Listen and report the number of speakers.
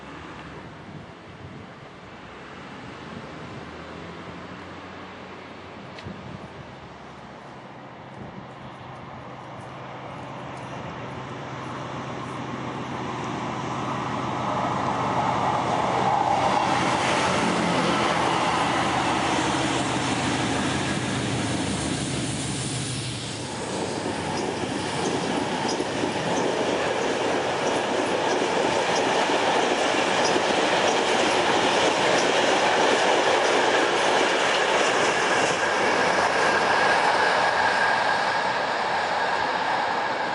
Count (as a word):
zero